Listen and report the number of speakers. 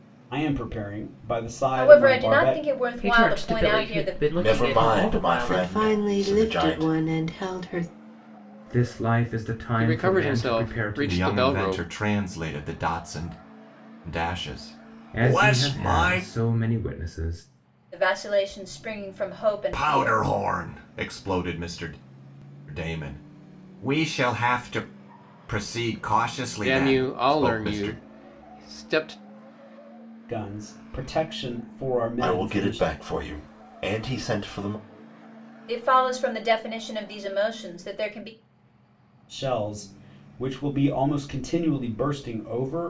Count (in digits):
8